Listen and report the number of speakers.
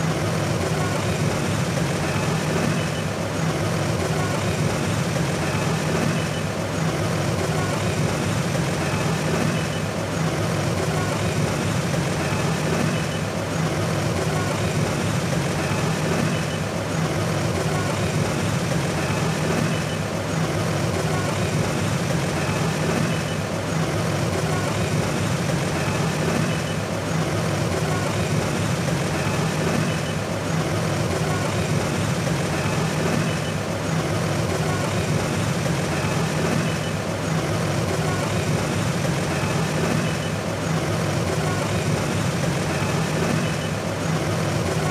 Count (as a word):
zero